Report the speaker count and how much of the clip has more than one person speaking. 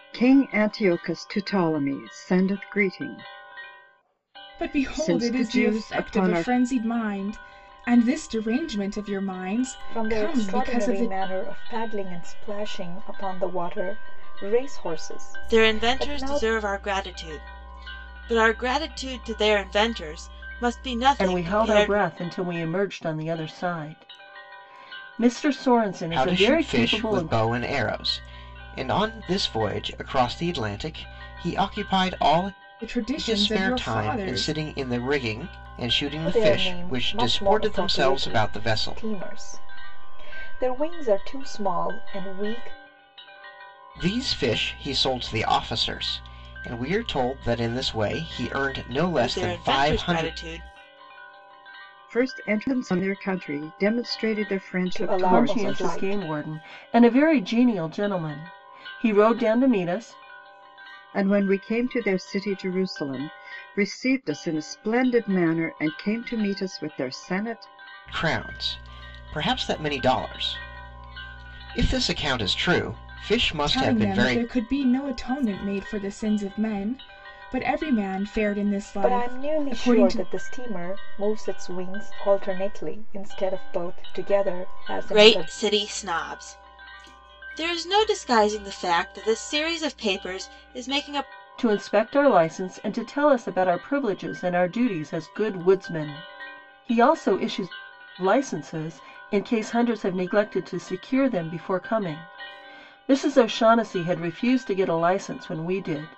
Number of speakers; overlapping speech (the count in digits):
6, about 15%